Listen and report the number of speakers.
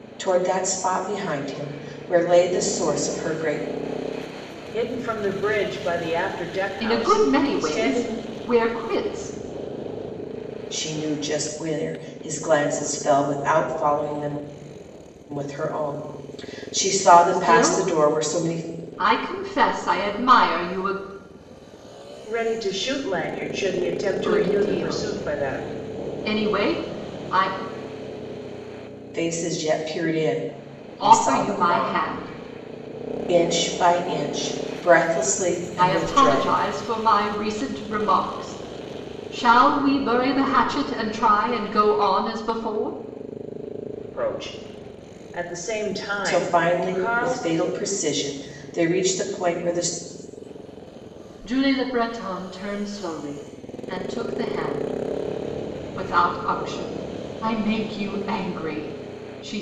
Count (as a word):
three